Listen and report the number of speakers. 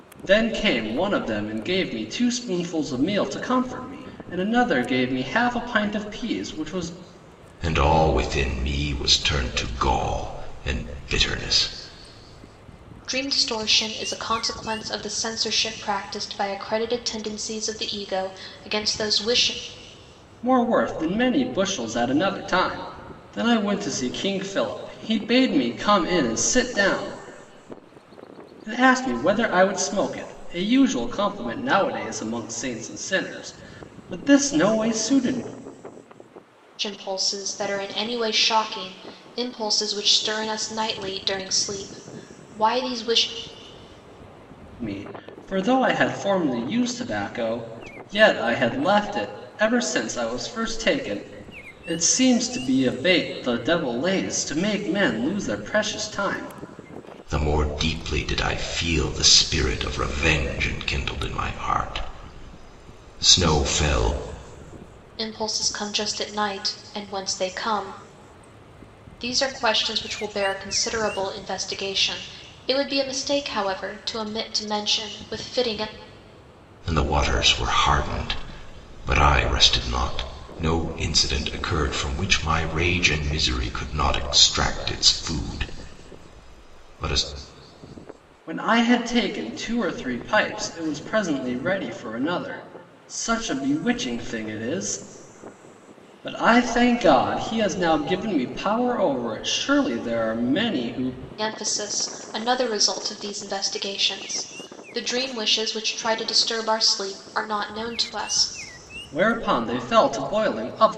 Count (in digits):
3